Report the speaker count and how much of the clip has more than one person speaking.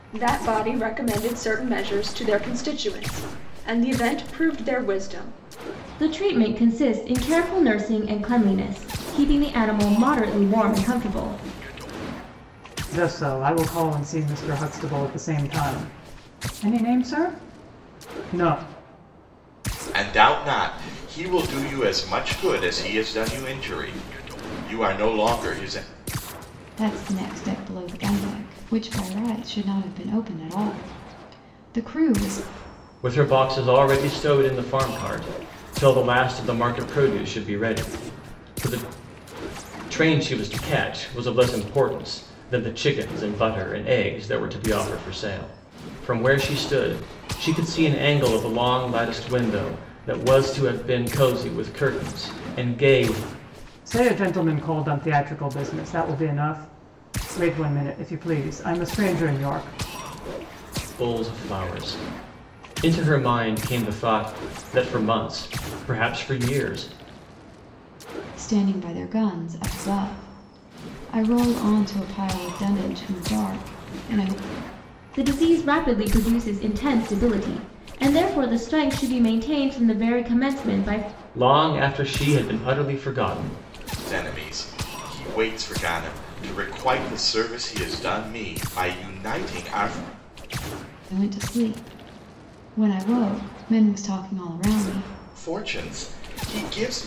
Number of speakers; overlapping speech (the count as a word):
six, no overlap